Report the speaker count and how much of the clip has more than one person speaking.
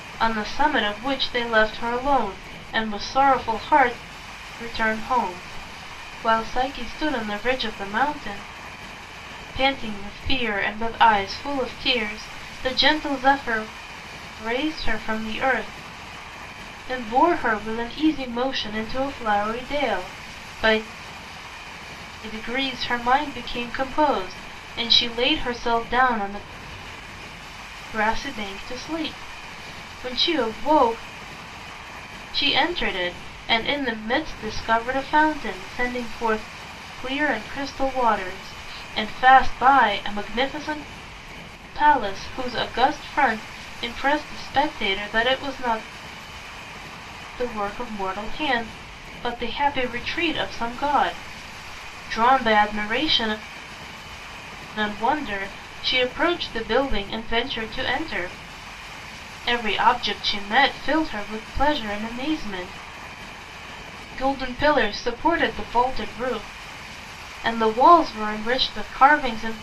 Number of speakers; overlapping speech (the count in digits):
1, no overlap